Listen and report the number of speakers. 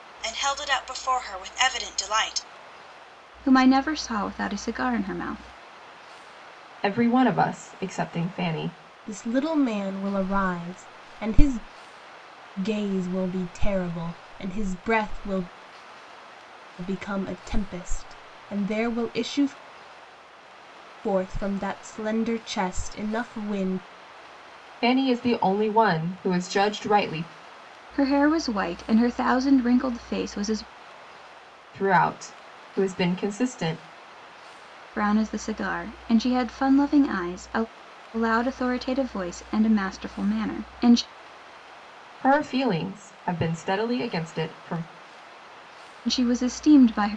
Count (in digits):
4